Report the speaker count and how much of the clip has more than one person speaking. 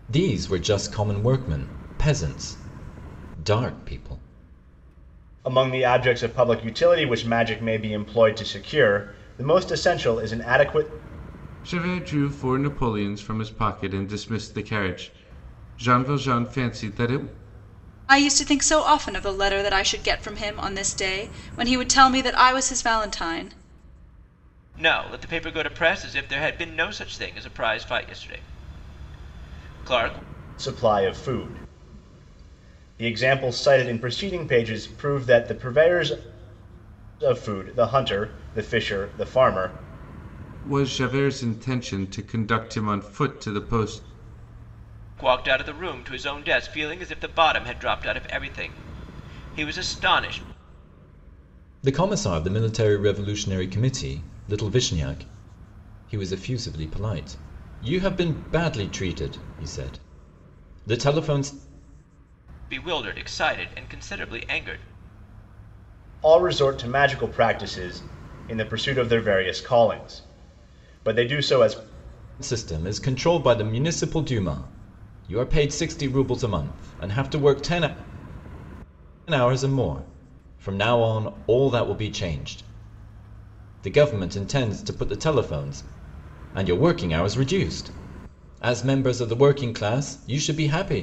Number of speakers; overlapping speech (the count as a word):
five, no overlap